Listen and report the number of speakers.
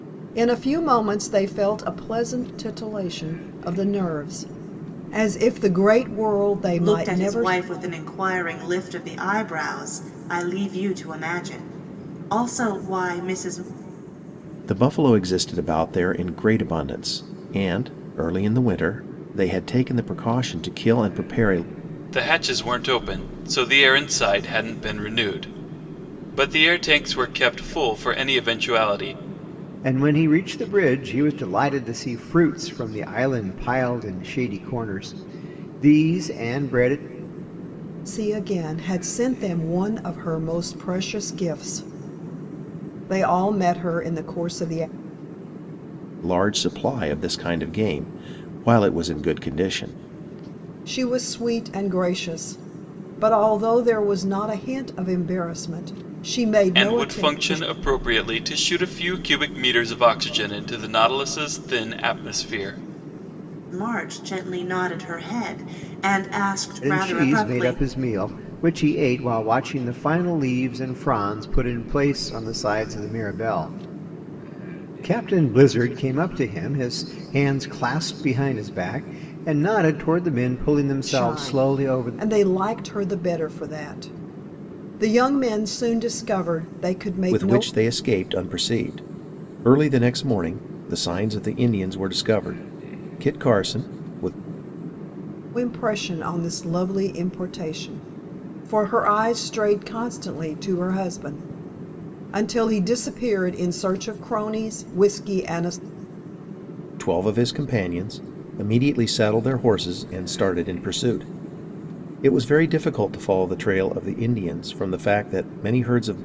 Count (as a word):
five